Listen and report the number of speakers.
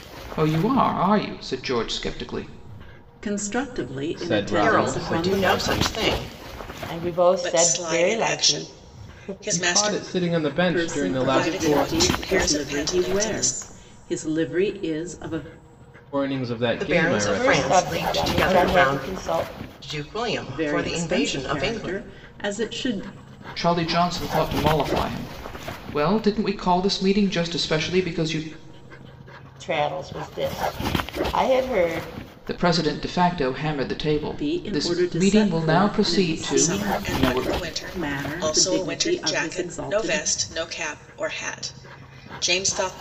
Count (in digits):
6